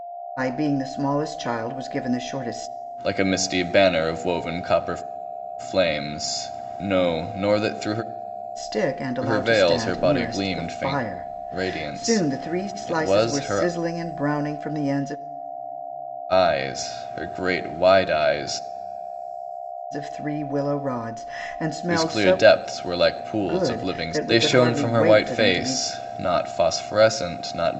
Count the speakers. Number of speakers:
two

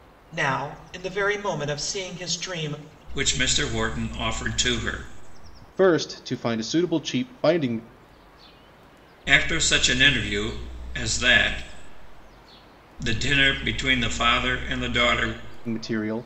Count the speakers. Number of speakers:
three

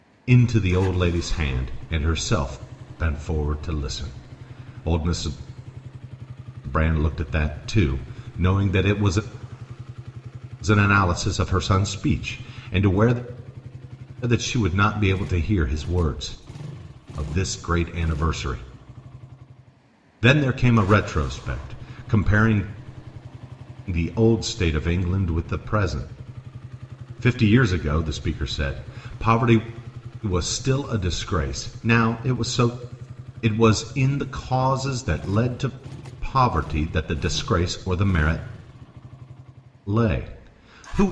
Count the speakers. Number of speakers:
one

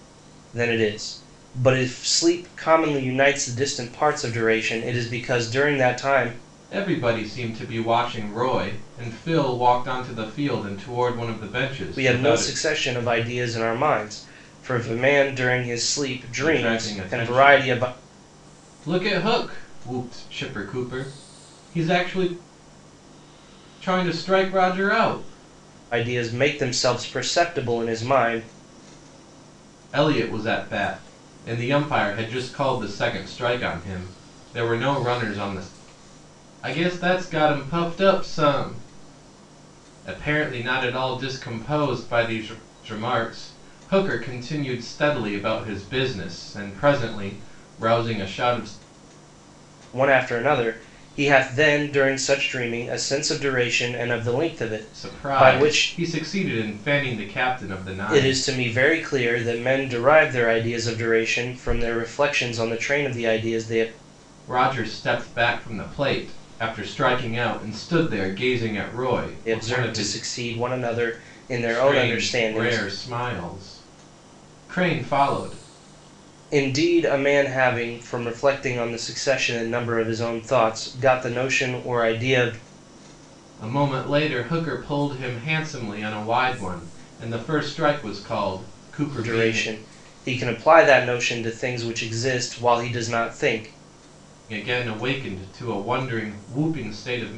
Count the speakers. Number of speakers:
two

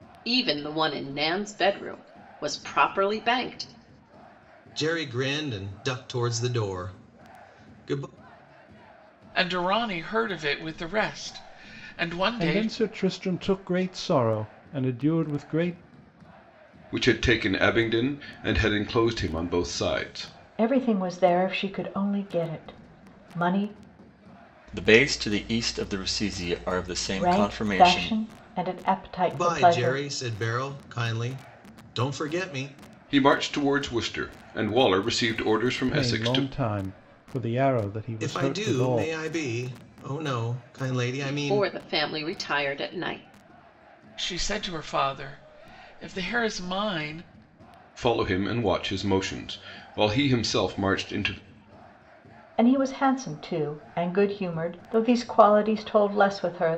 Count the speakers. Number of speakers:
seven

